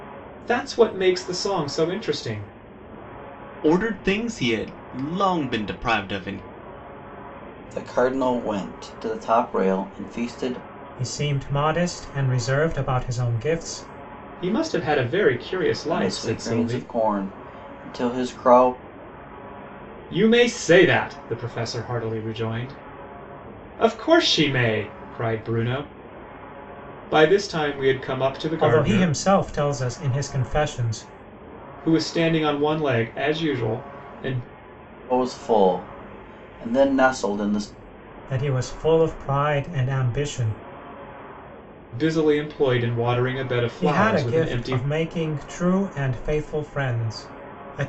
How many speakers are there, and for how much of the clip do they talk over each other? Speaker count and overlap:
four, about 6%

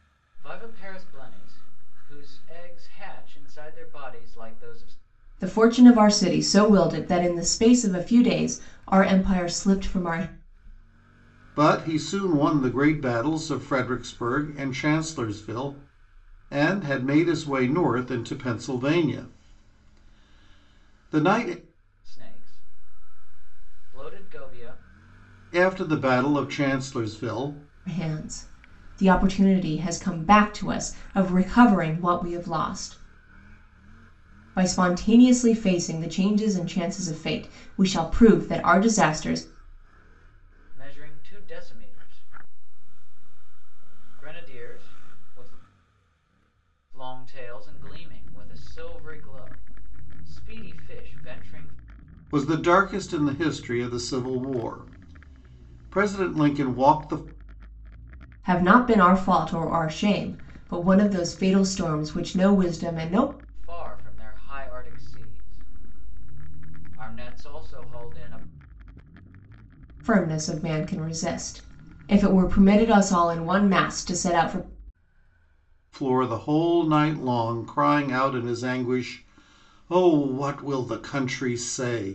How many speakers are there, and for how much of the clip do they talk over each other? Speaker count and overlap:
three, no overlap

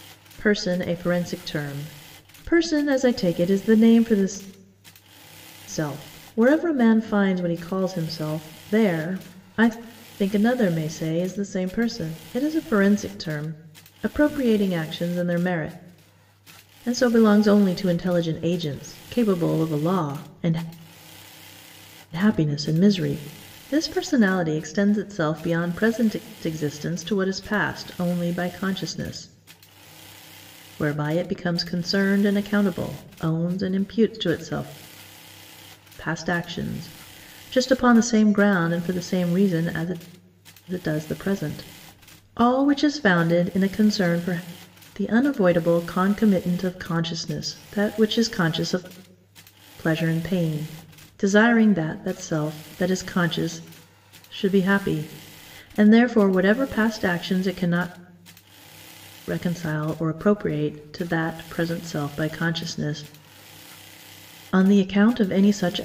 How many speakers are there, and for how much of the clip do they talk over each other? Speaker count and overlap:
one, no overlap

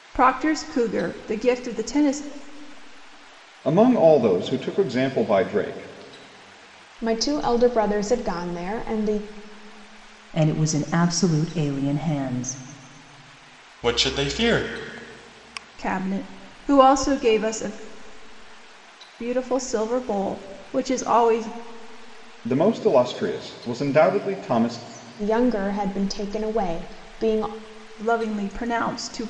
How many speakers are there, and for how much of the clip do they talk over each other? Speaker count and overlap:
five, no overlap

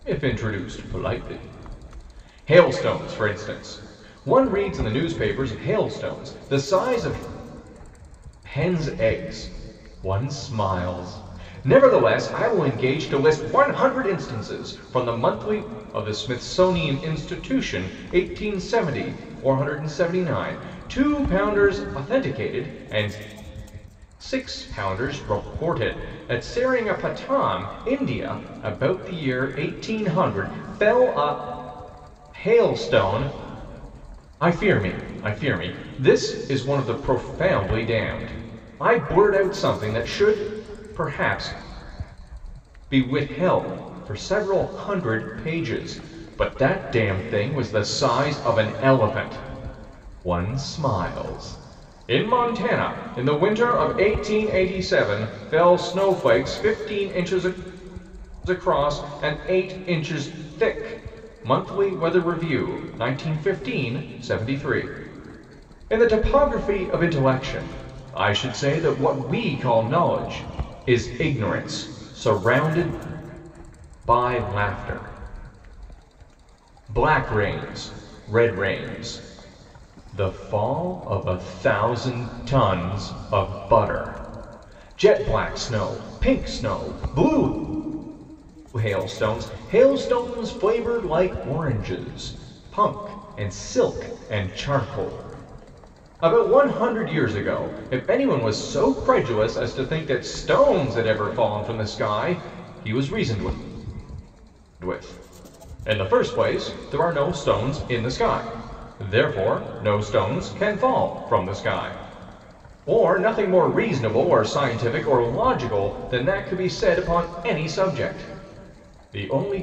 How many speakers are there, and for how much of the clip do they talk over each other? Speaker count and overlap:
one, no overlap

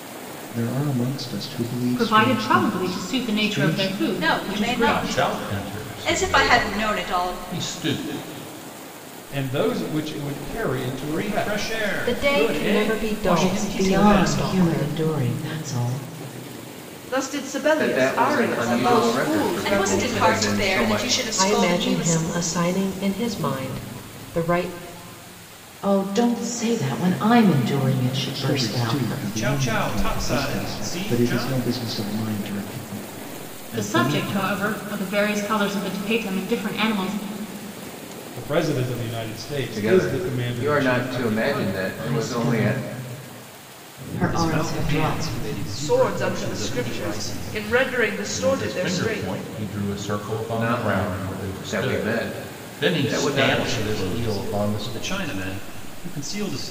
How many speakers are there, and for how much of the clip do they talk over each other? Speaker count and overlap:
ten, about 51%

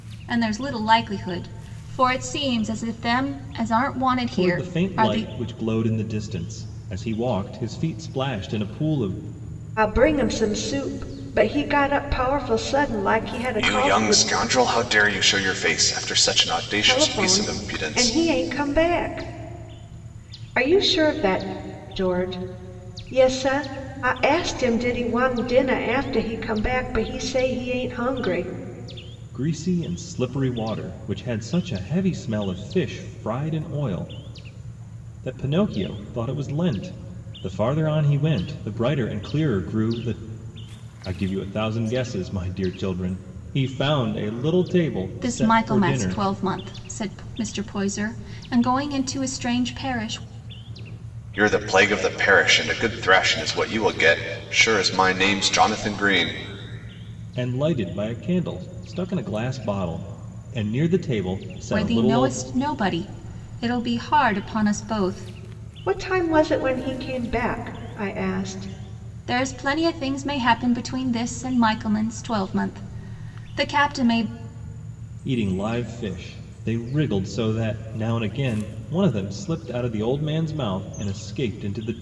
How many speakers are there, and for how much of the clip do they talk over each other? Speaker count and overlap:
four, about 6%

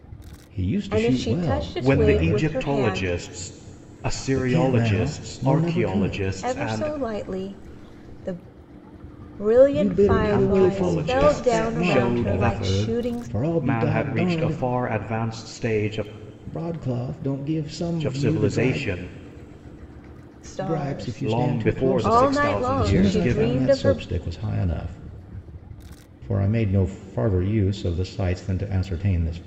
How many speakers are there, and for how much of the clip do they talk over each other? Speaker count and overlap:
three, about 47%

